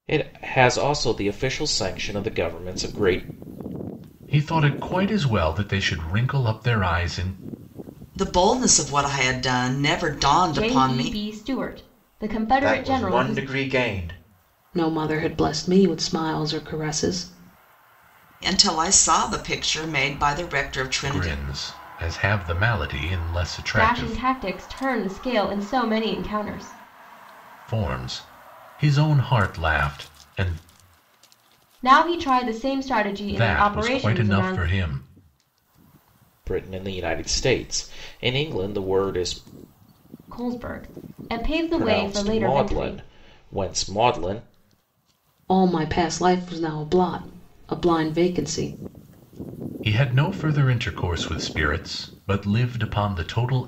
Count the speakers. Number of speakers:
six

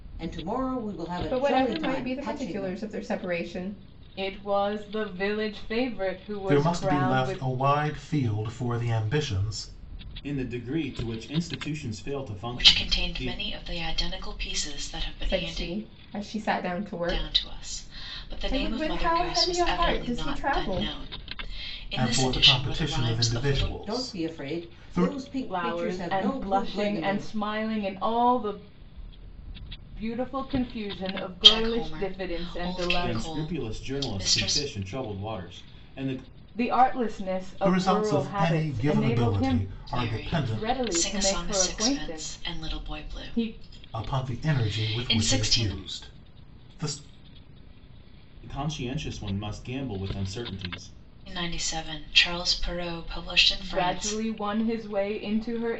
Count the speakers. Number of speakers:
six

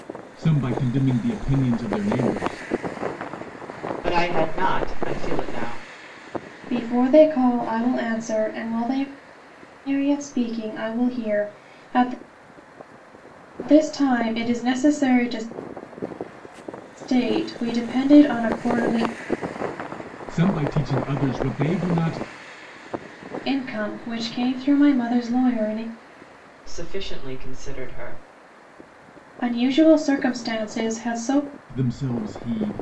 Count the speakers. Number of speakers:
three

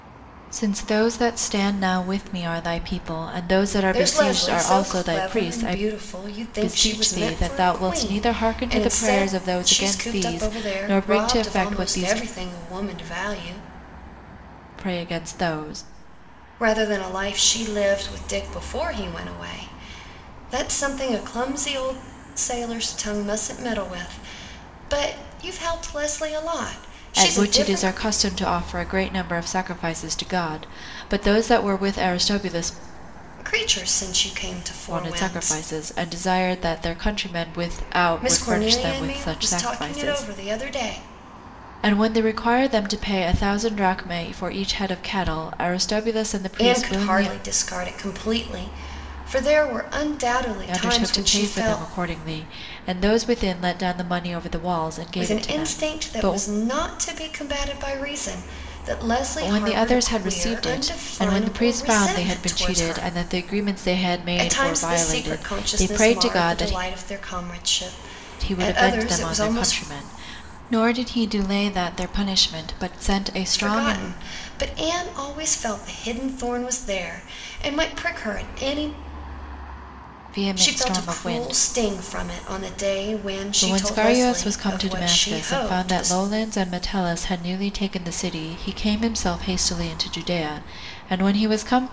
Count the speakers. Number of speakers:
two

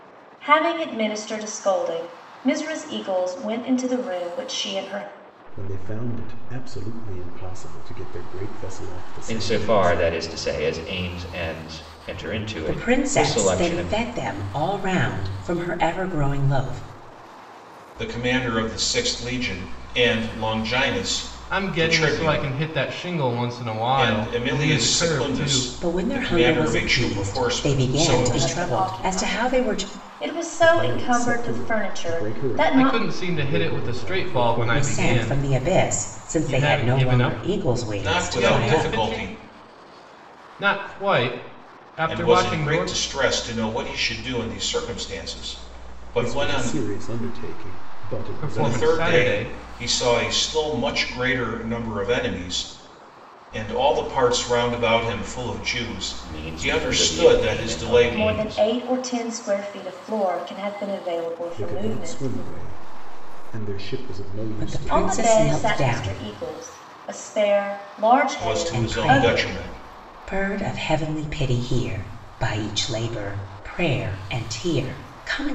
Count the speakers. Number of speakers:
six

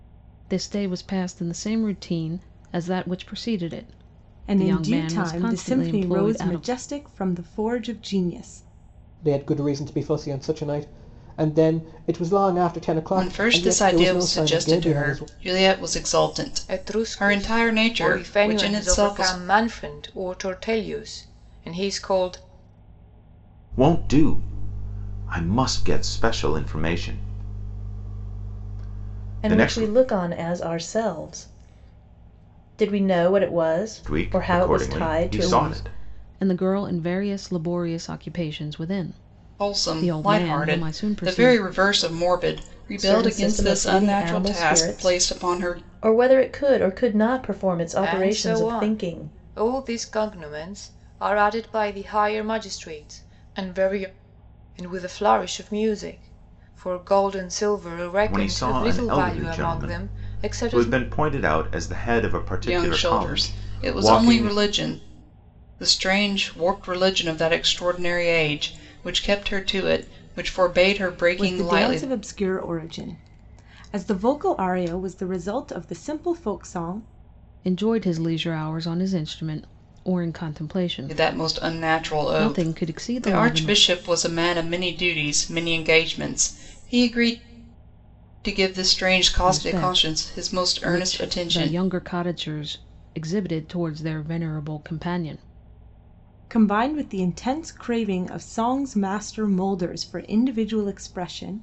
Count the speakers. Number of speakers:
seven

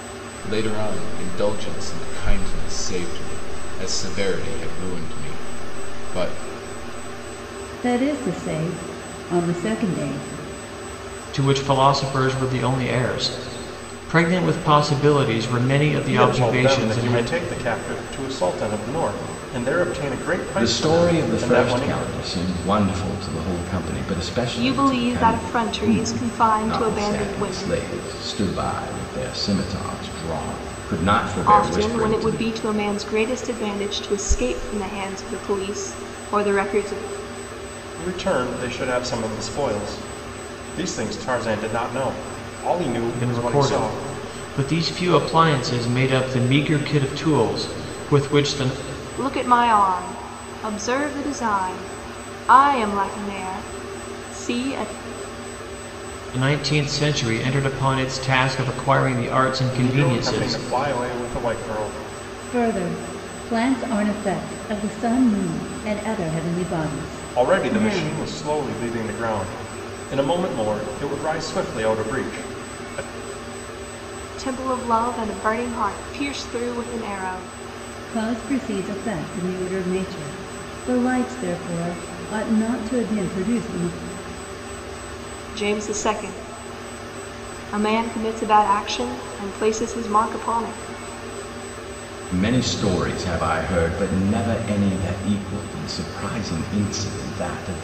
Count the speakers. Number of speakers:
six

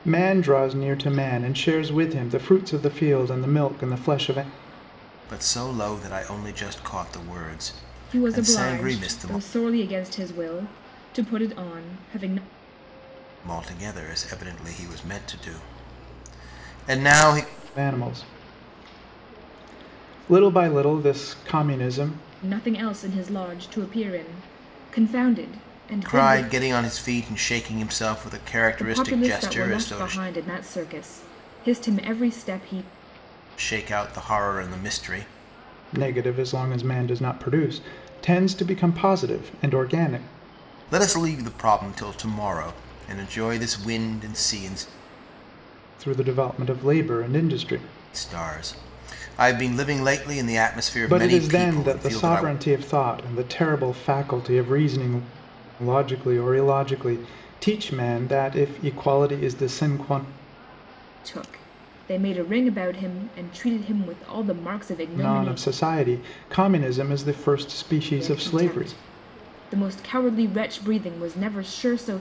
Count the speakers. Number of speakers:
three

